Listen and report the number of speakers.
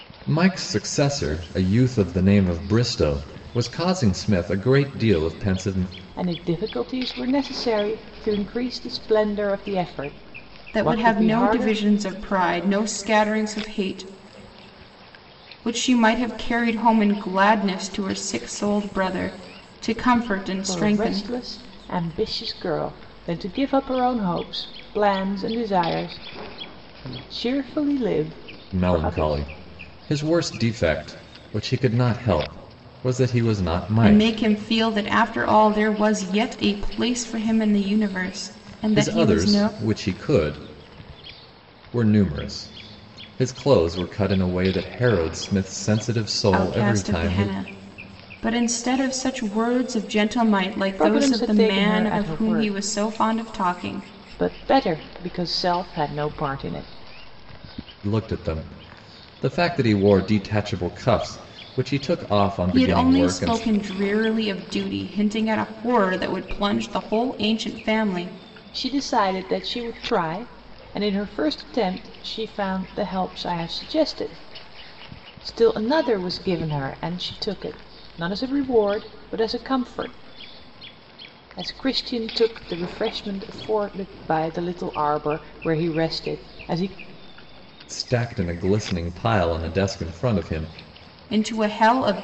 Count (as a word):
three